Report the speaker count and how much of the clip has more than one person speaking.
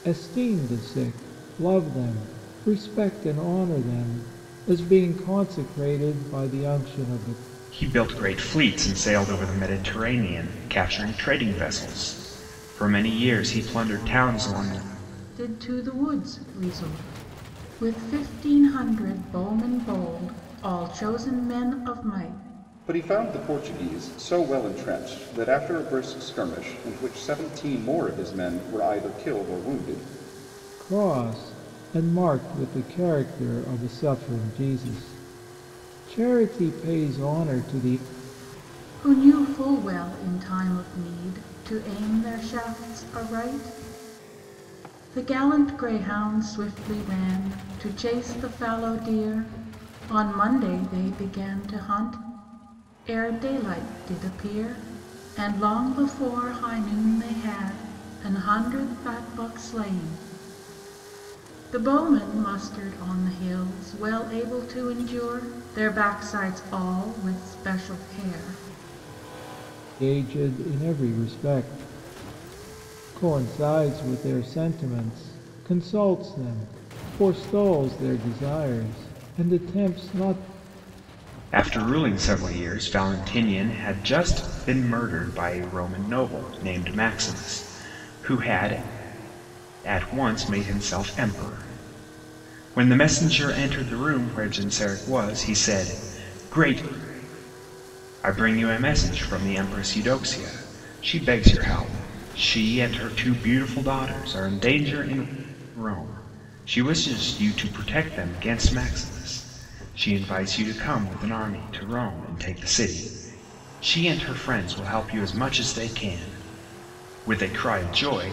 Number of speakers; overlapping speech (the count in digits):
4, no overlap